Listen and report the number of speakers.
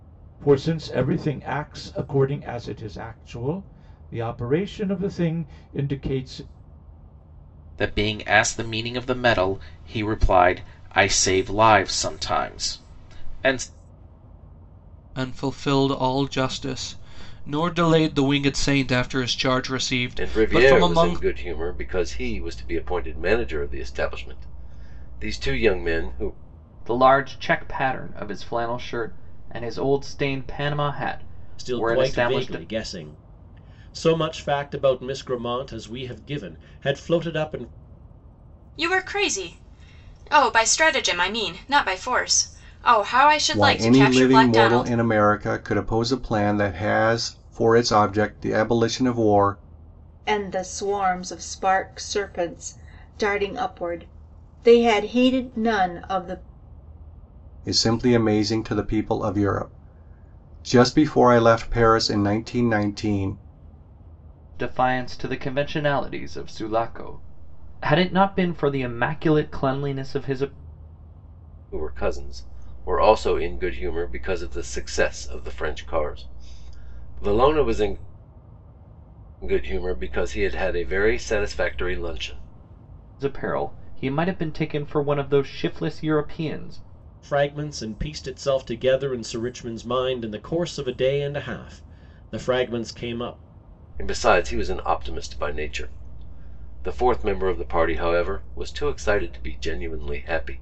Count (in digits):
9